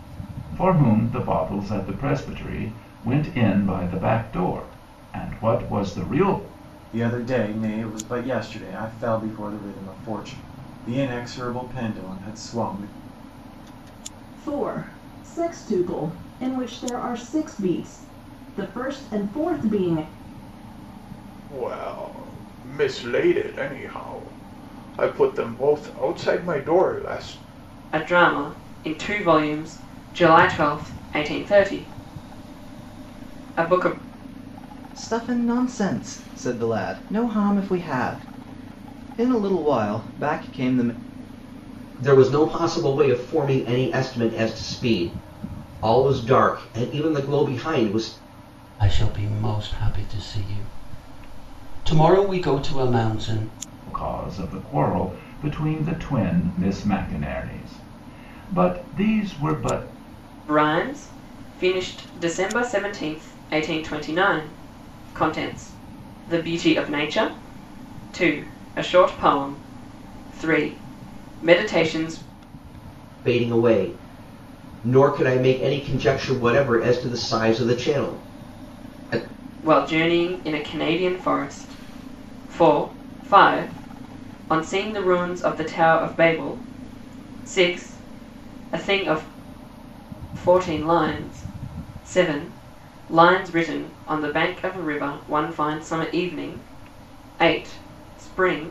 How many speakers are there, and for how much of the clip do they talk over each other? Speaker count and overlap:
8, no overlap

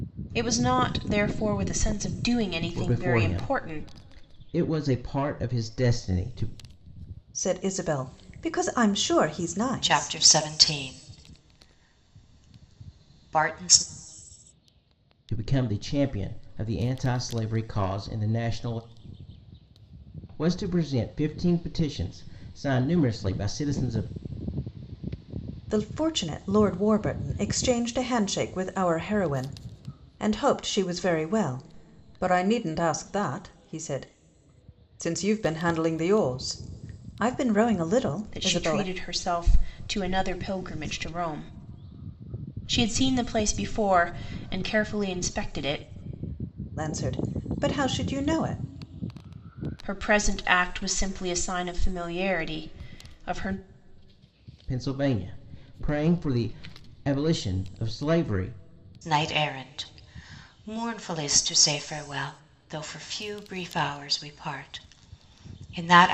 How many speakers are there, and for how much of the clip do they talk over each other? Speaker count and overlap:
4, about 4%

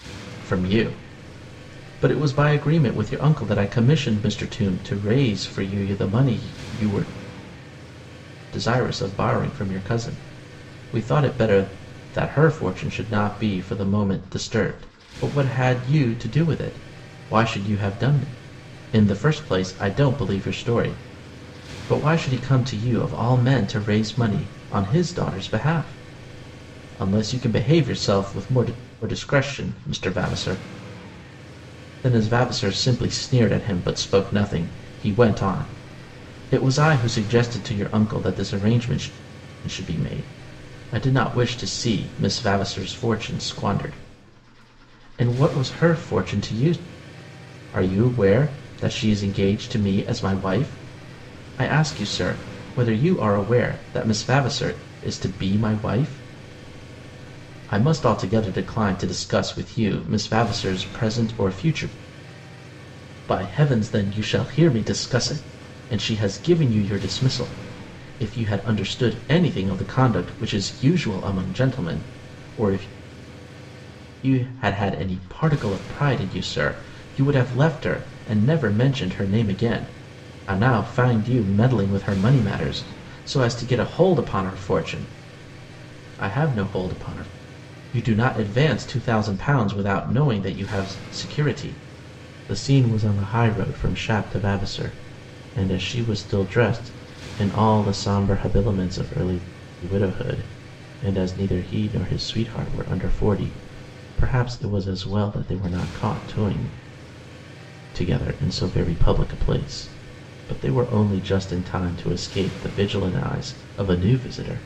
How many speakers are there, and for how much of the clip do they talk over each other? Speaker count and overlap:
1, no overlap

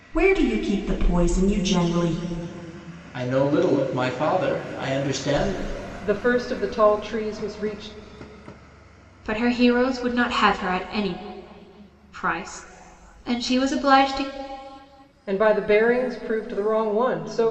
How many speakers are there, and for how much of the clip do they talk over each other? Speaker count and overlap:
4, no overlap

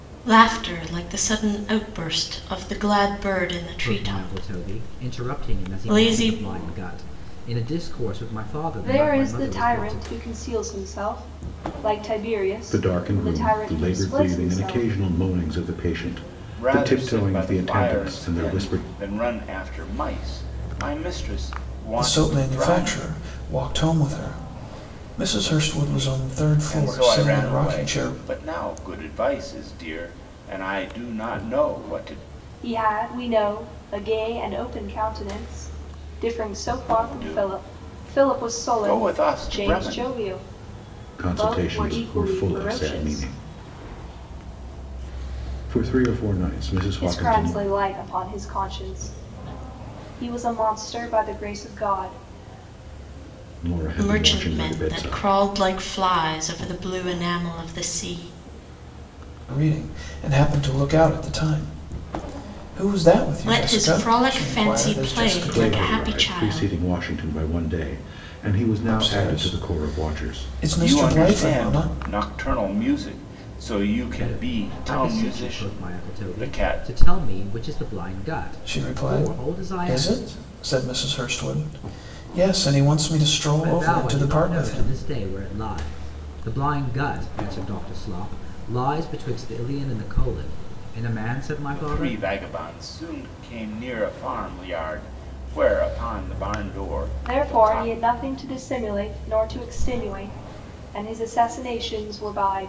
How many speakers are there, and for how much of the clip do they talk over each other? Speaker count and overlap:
6, about 31%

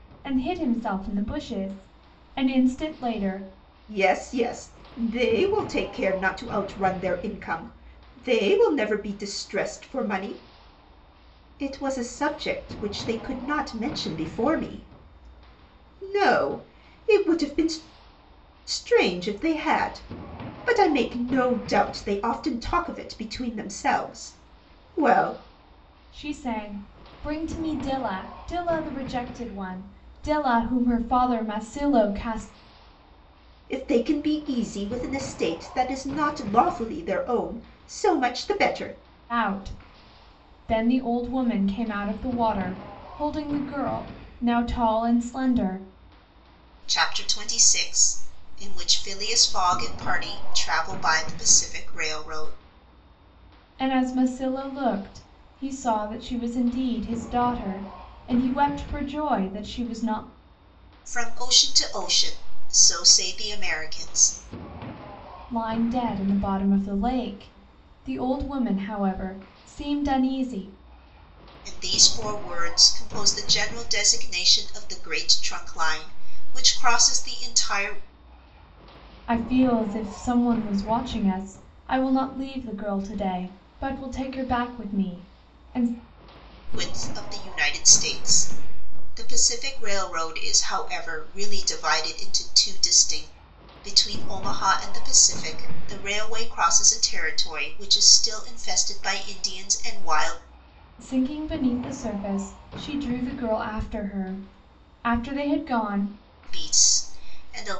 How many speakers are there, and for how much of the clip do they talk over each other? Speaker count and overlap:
2, no overlap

